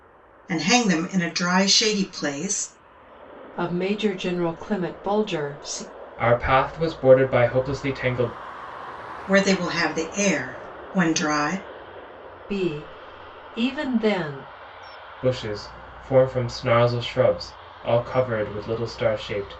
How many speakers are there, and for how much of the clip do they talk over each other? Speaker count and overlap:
3, no overlap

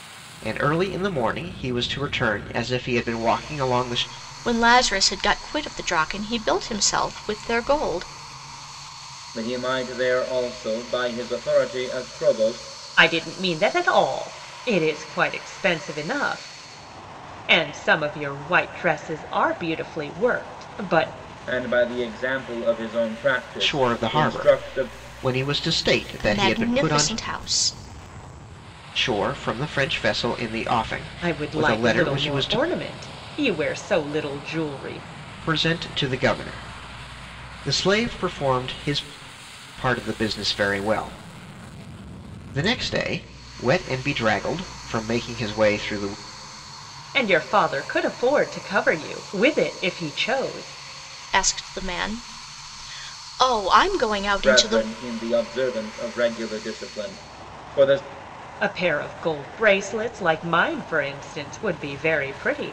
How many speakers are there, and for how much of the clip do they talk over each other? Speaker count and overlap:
4, about 7%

